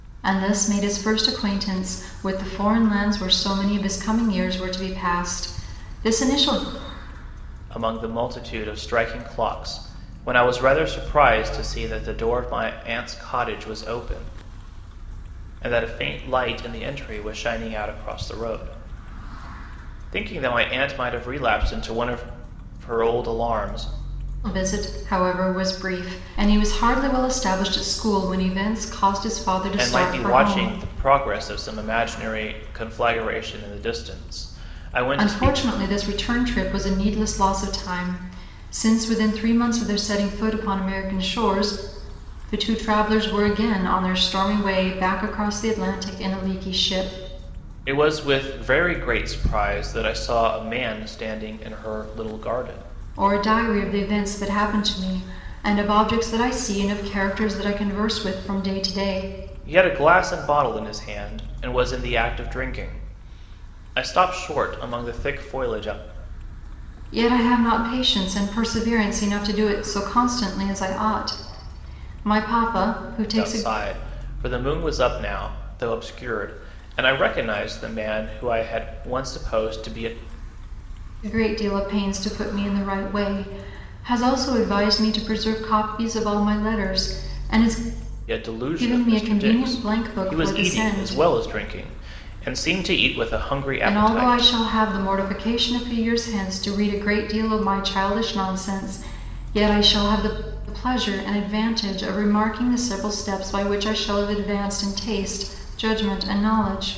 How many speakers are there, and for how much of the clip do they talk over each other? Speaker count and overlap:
2, about 5%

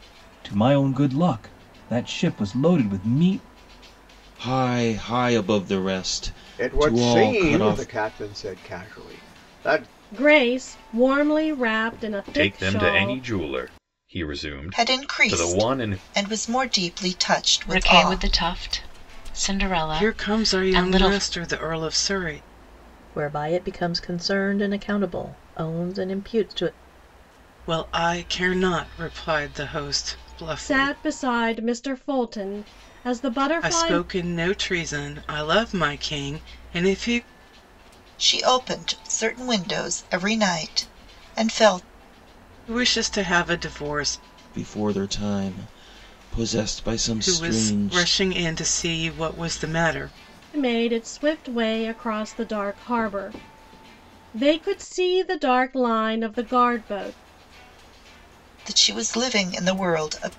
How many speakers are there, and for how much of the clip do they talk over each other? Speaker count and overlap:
9, about 12%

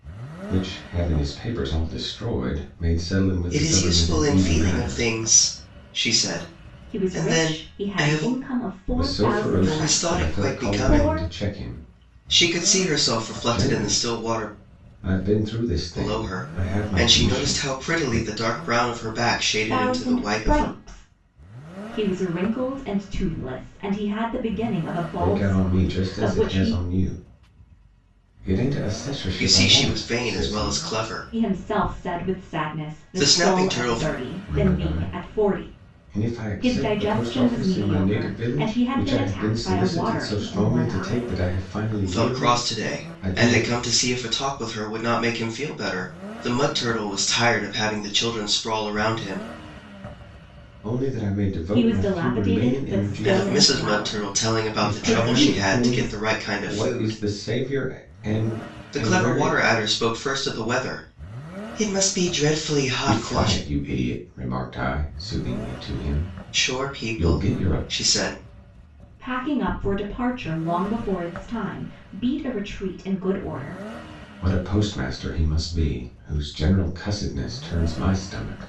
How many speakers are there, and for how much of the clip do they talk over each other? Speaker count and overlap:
3, about 41%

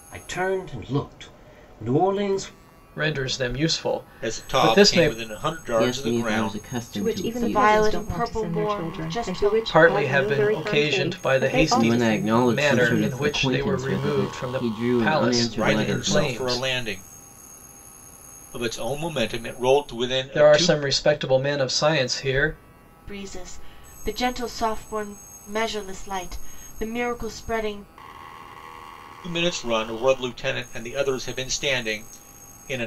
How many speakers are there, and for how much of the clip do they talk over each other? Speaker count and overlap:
6, about 37%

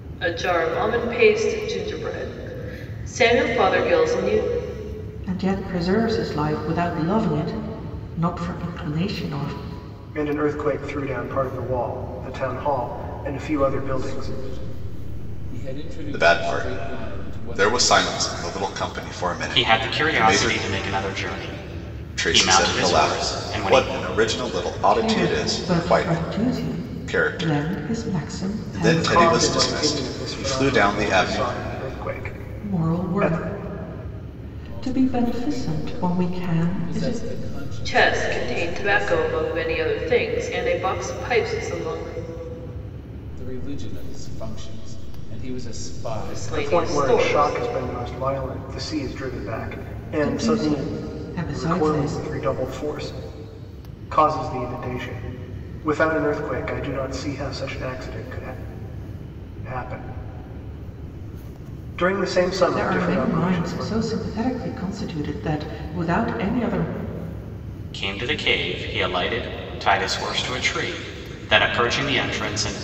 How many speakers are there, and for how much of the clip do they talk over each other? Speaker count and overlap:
6, about 28%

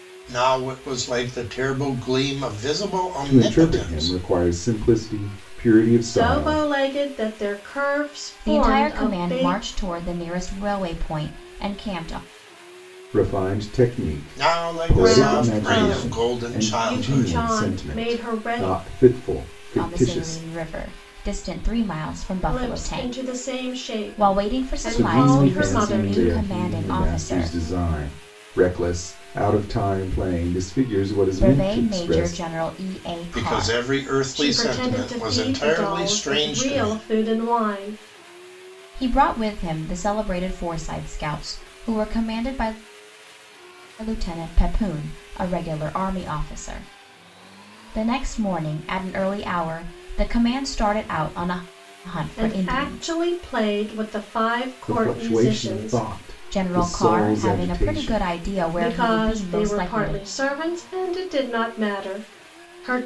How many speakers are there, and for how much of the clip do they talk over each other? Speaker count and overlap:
4, about 35%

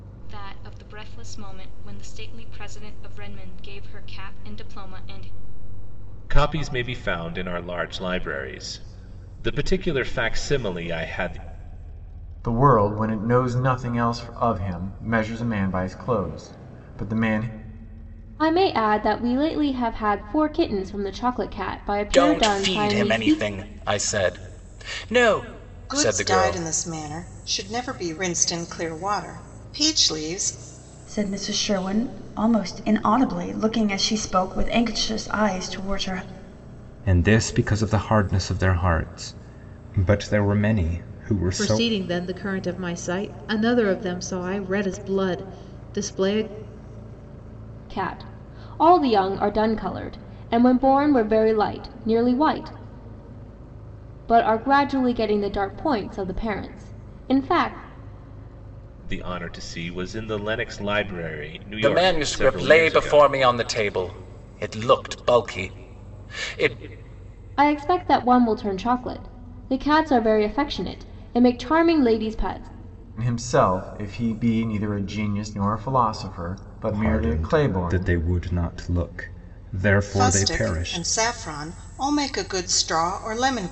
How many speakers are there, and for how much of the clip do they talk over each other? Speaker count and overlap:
9, about 7%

